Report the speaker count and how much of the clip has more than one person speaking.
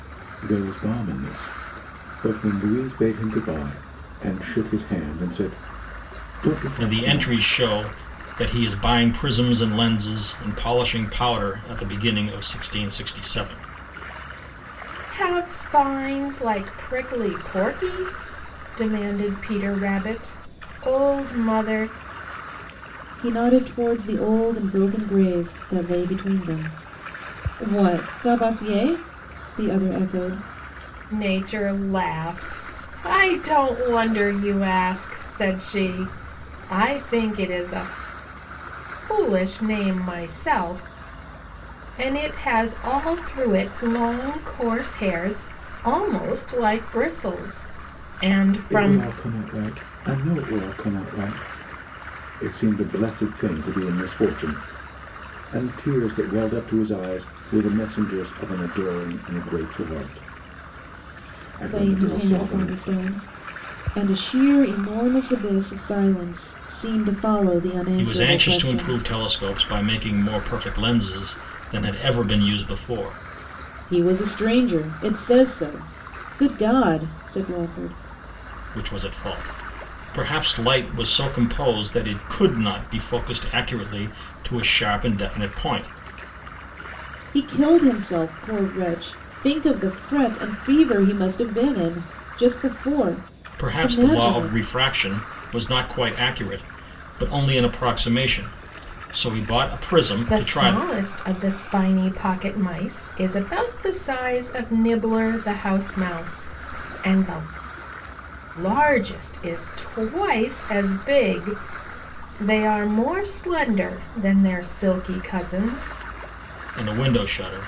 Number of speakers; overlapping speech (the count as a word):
four, about 4%